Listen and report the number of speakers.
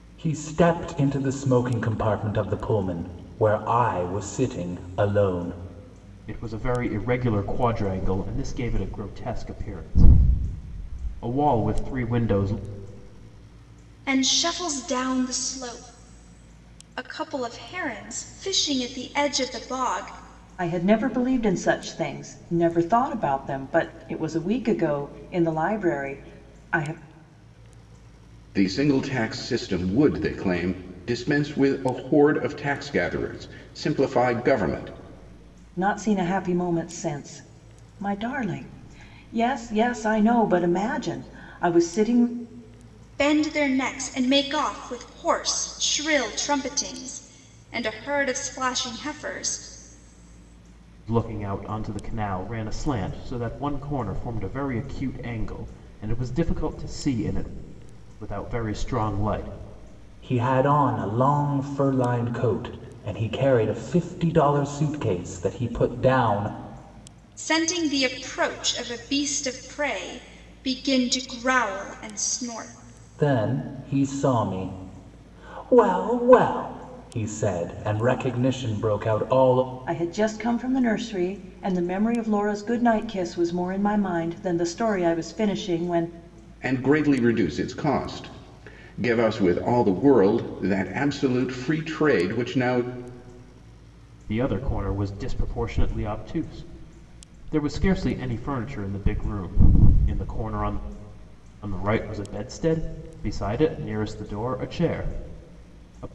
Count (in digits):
5